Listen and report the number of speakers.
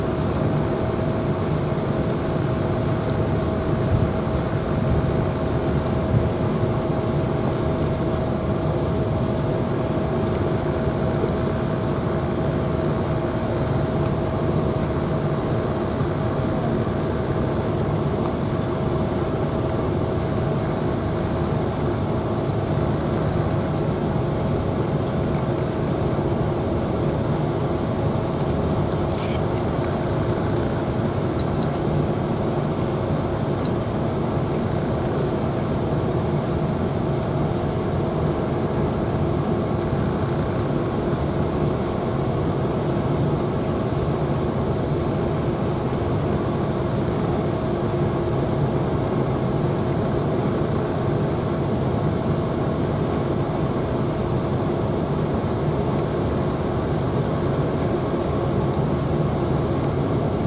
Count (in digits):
0